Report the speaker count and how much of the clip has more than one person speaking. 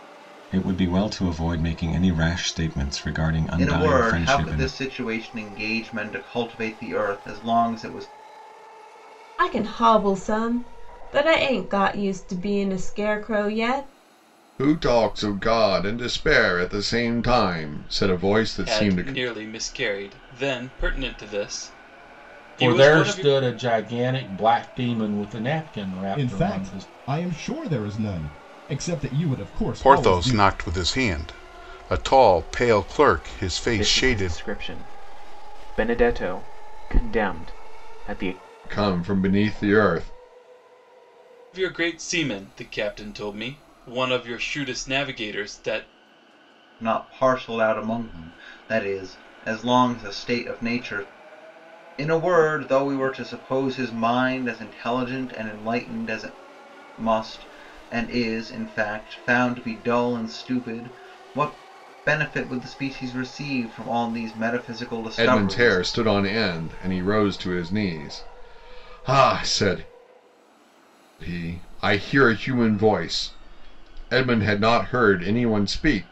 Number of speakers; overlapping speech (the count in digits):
9, about 7%